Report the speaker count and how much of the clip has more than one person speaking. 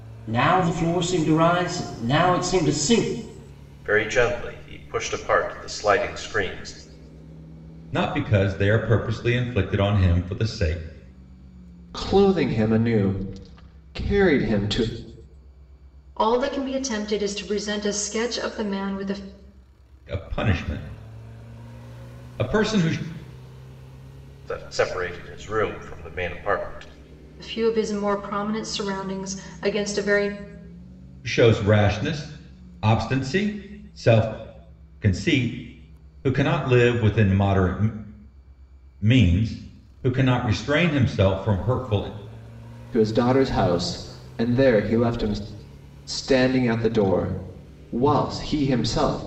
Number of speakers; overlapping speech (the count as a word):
five, no overlap